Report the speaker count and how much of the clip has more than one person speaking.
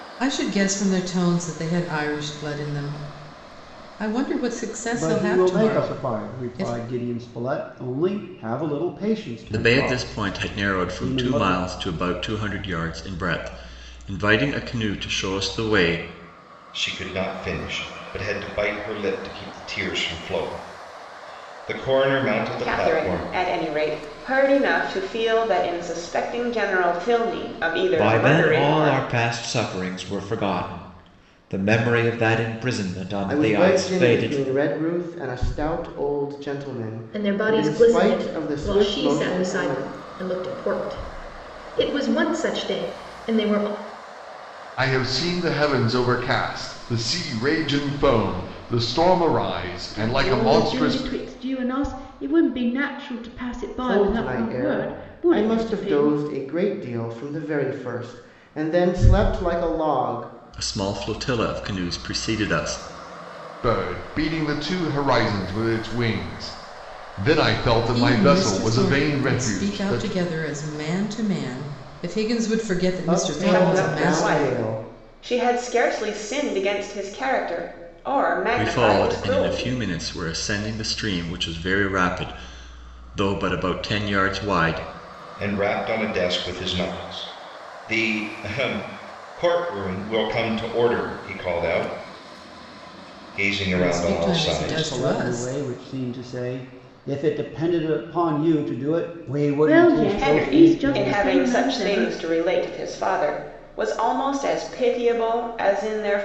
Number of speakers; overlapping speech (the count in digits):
10, about 22%